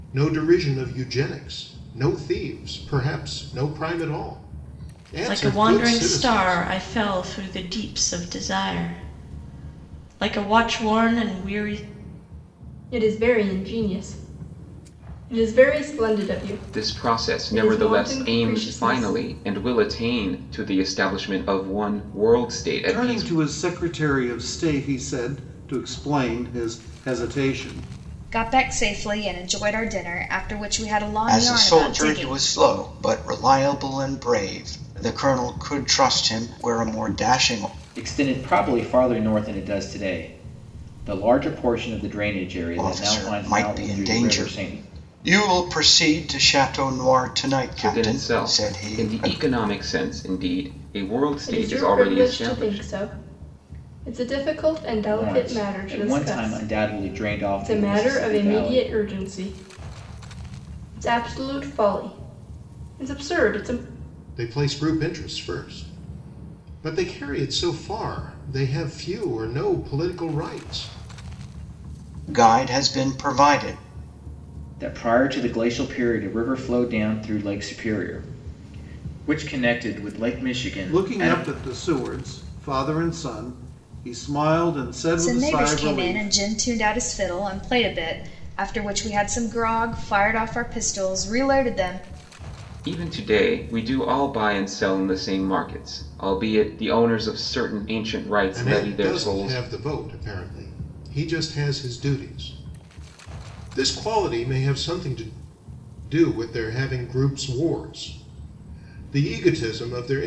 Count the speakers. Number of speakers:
eight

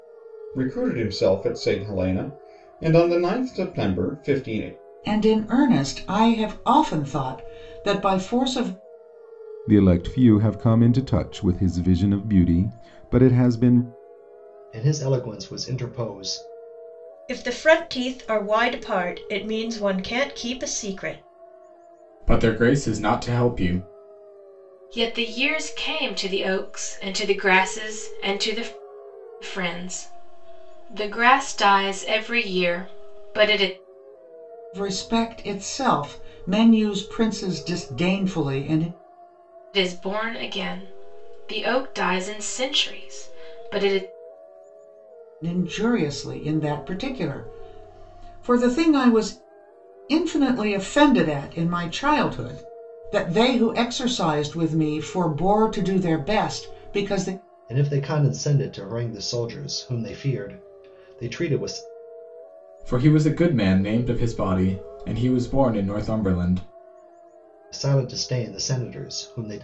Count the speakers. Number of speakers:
seven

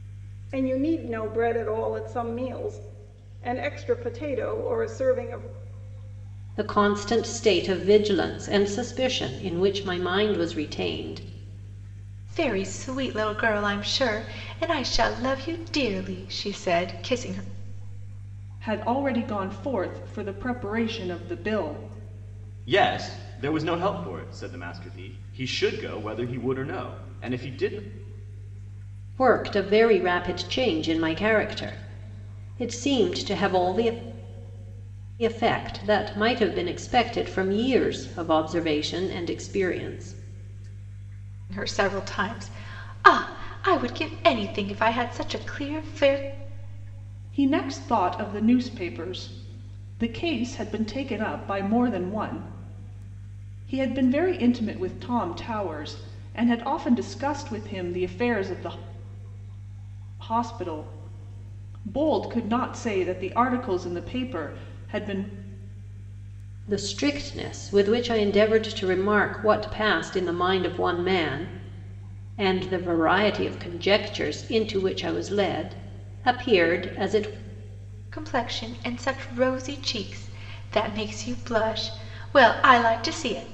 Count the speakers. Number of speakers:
five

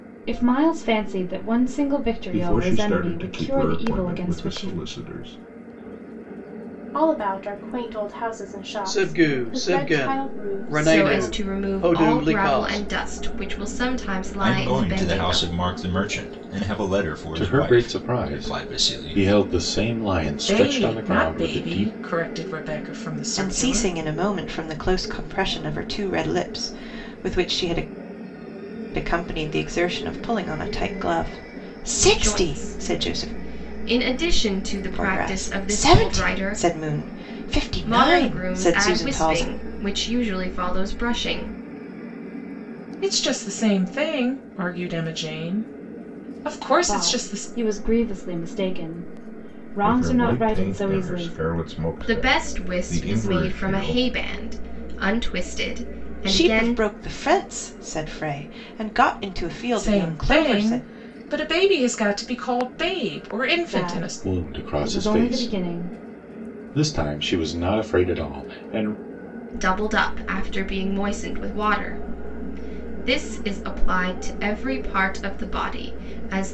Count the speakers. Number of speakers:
nine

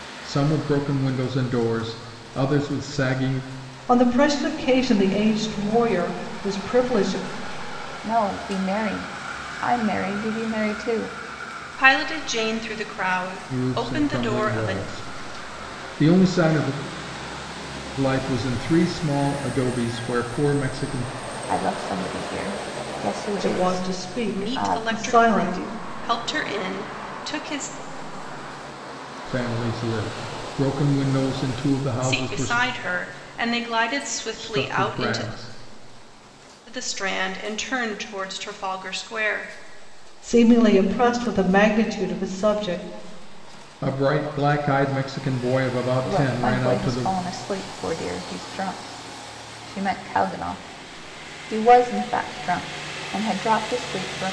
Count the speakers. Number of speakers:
four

